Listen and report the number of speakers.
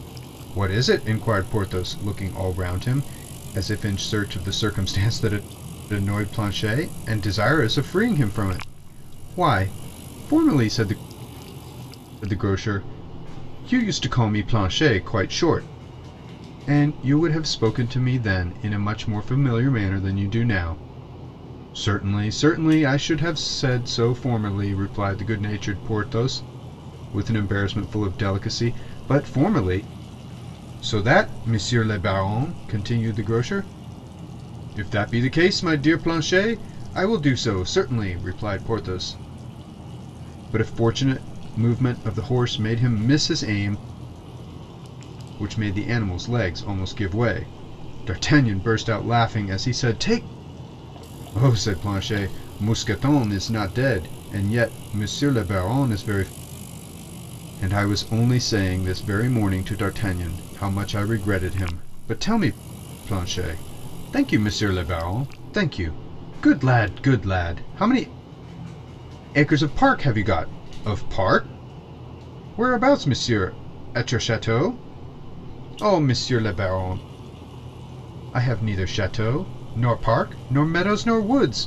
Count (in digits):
1